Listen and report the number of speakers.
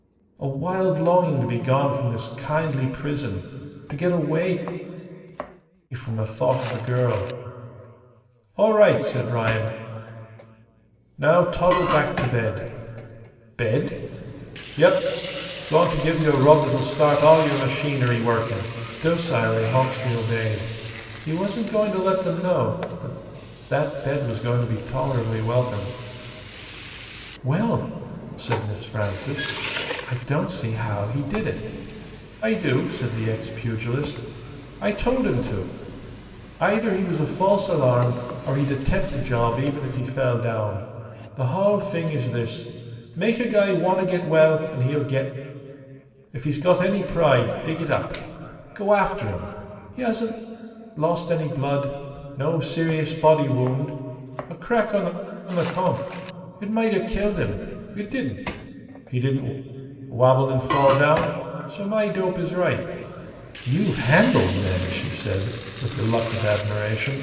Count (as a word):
one